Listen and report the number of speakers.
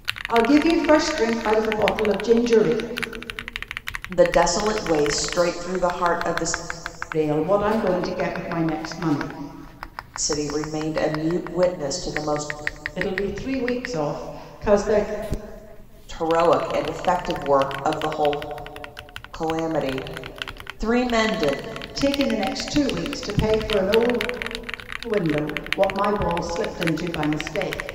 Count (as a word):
two